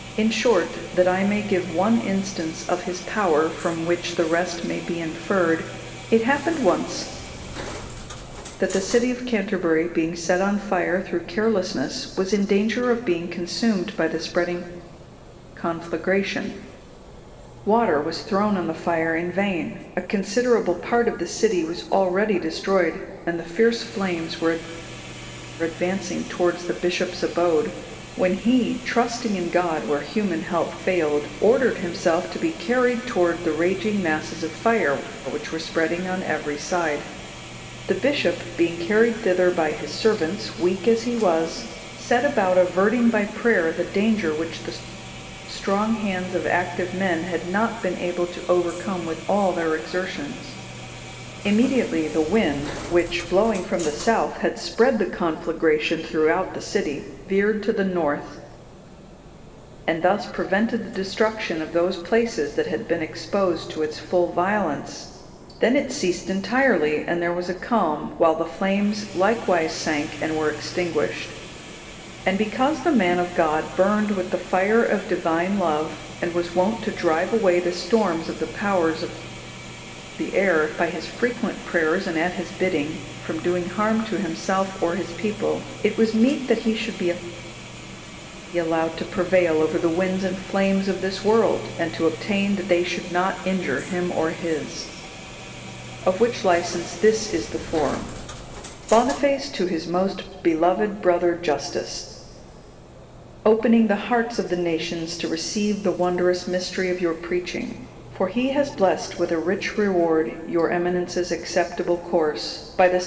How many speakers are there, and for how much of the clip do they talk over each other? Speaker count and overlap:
1, no overlap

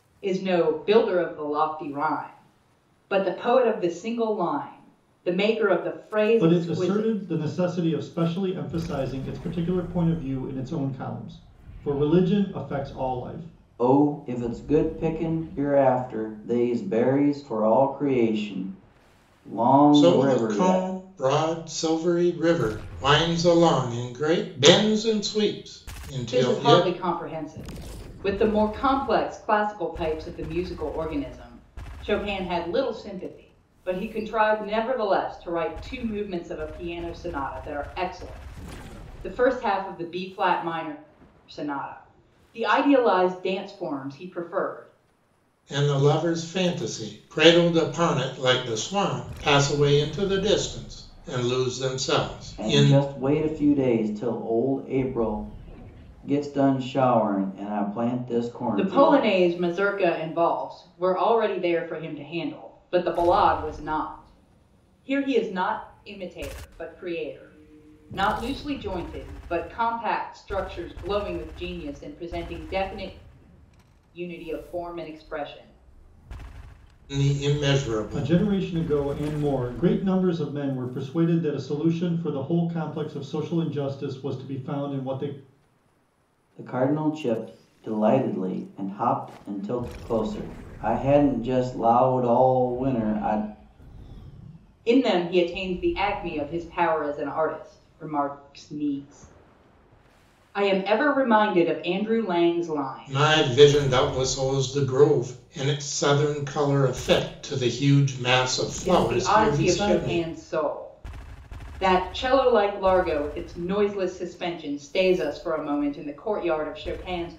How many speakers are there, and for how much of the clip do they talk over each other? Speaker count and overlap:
4, about 5%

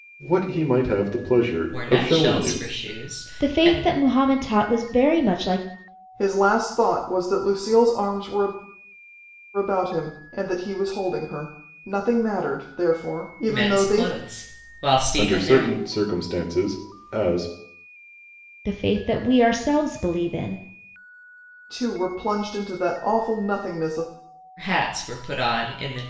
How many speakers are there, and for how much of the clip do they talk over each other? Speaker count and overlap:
4, about 11%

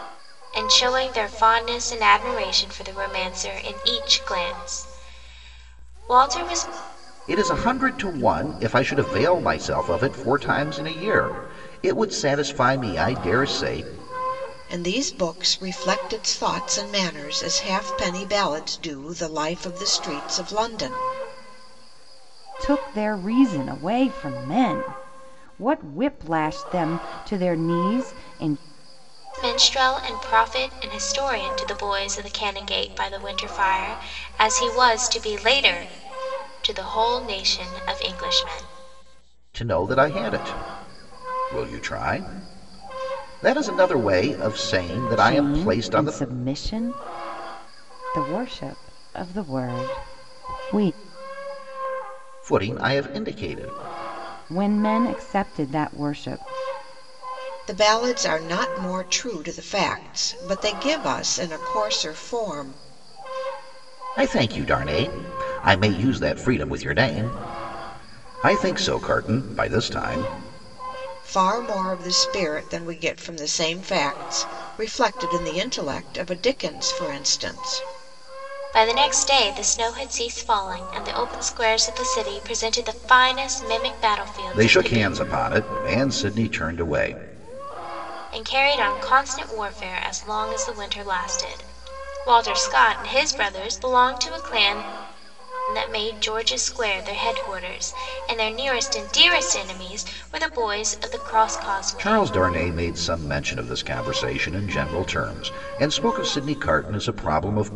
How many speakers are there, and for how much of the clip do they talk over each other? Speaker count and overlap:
4, about 2%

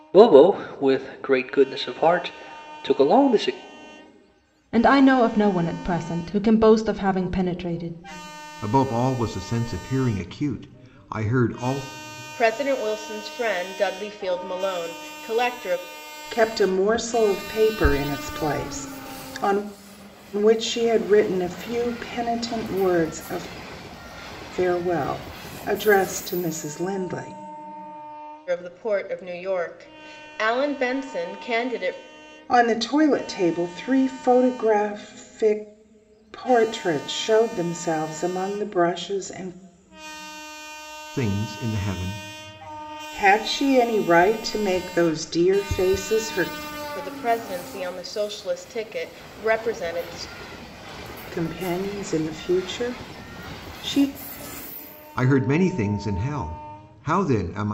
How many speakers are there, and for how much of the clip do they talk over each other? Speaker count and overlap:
5, no overlap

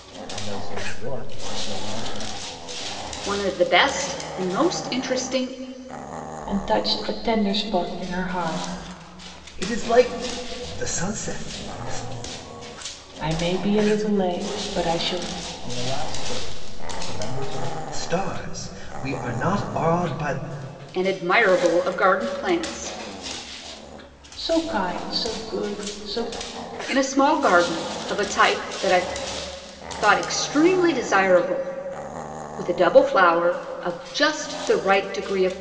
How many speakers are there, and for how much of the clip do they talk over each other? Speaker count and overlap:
4, no overlap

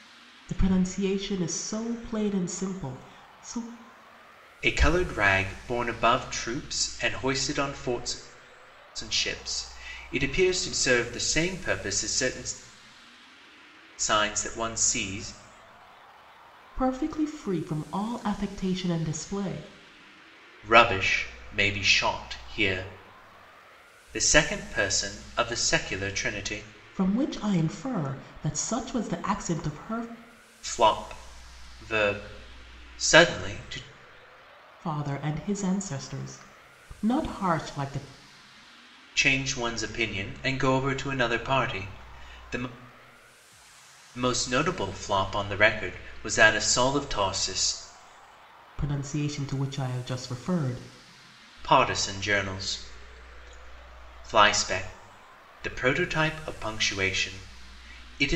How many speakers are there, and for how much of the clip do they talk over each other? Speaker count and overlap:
2, no overlap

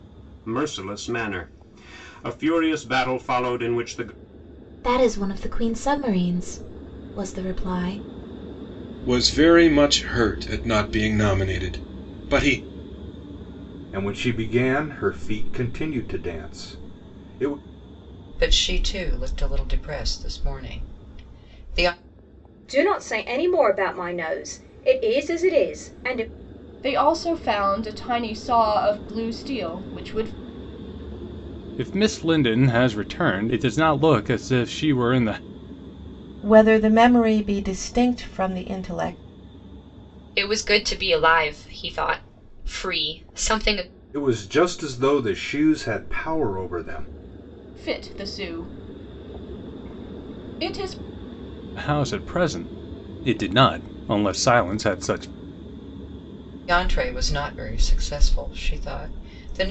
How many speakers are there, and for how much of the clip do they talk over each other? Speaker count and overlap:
10, no overlap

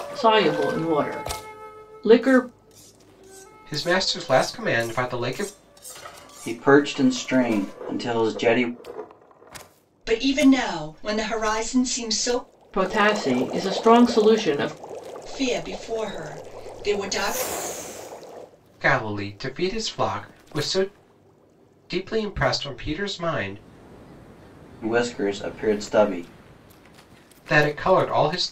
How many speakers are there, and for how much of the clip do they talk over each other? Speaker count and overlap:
4, no overlap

